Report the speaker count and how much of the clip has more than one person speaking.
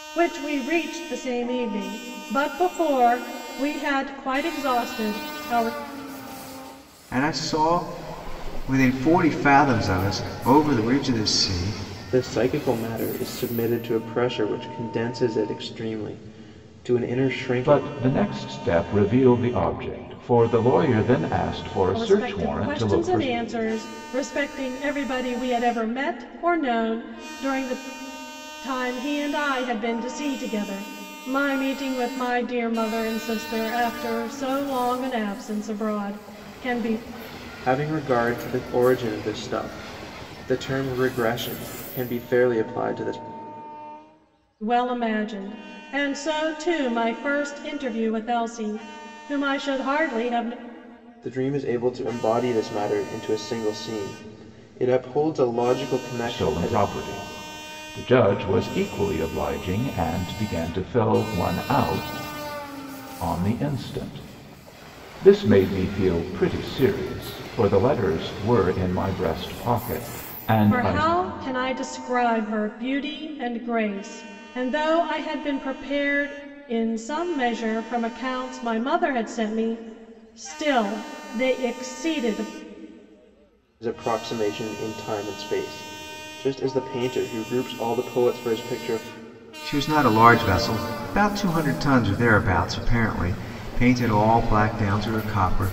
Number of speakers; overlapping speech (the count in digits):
4, about 3%